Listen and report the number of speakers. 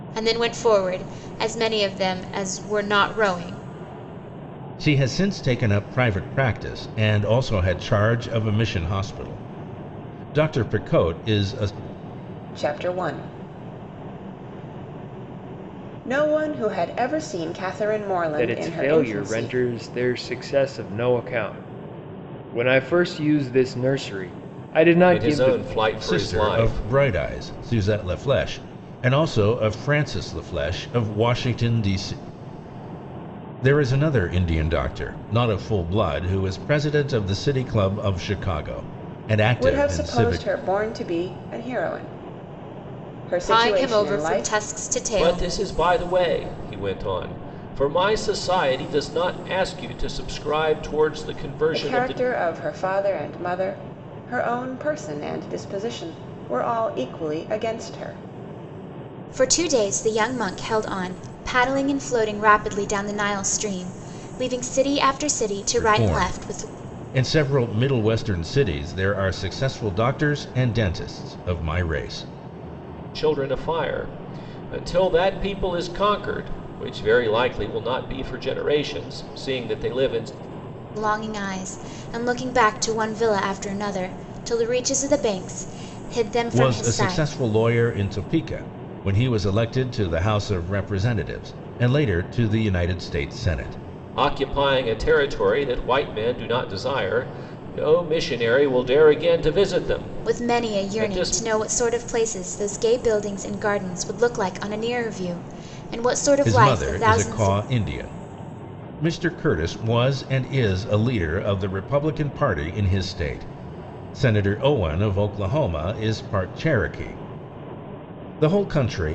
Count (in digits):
5